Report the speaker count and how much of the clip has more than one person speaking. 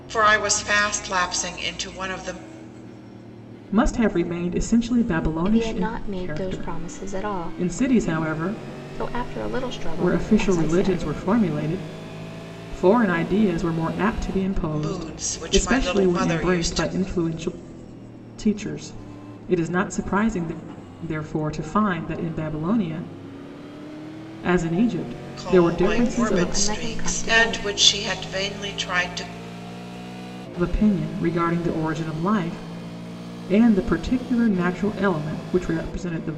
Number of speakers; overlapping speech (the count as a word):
three, about 20%